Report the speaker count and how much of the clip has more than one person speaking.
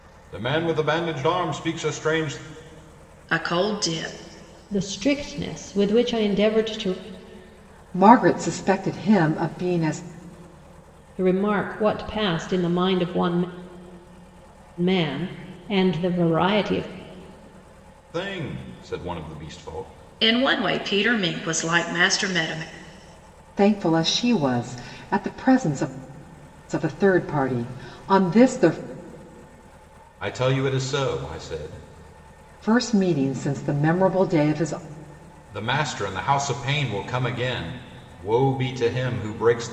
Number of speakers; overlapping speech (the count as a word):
four, no overlap